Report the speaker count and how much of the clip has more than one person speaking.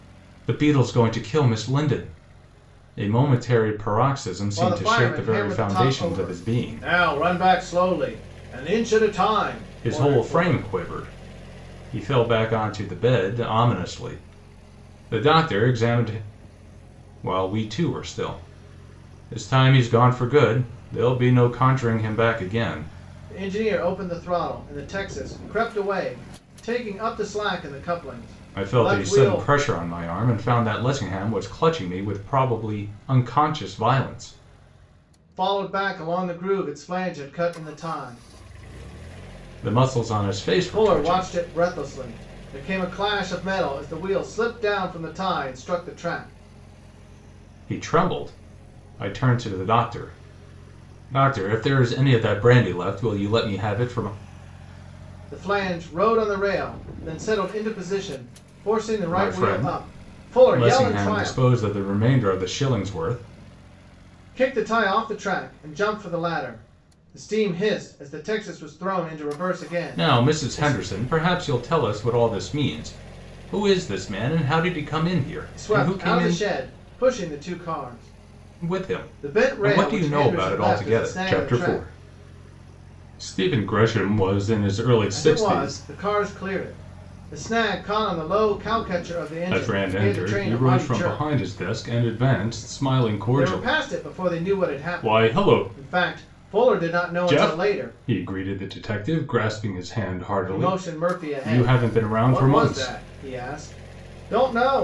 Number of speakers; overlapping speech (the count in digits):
2, about 19%